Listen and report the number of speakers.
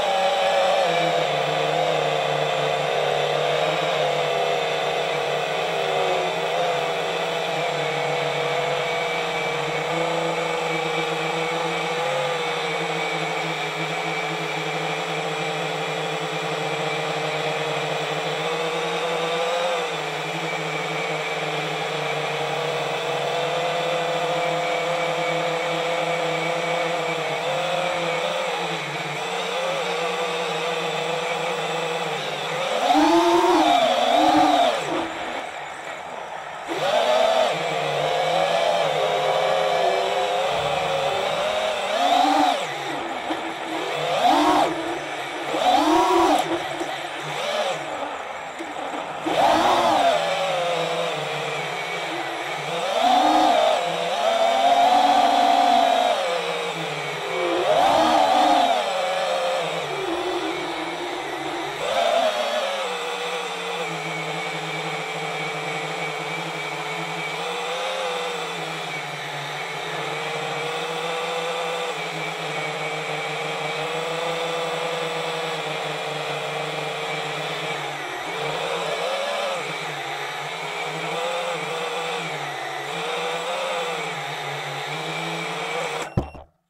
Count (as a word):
zero